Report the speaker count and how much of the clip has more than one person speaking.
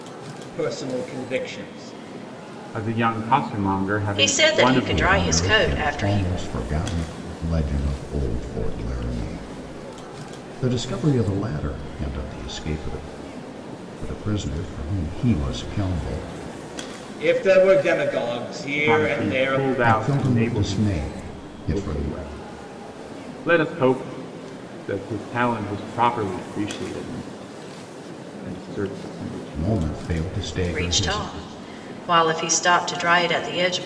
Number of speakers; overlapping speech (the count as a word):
four, about 18%